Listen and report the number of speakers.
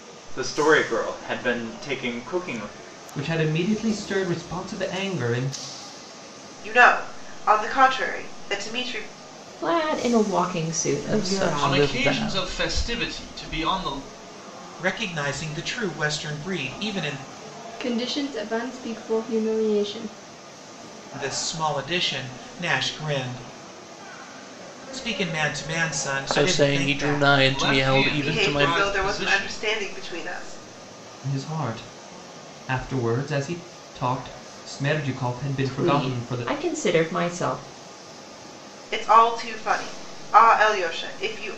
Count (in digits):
8